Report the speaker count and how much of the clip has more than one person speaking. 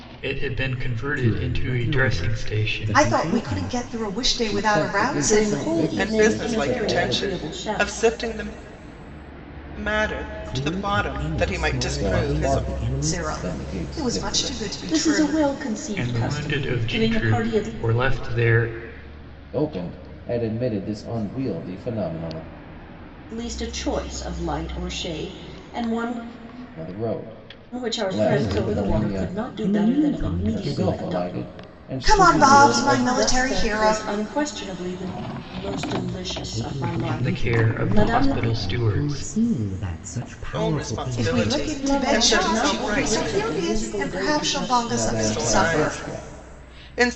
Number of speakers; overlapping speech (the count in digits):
6, about 57%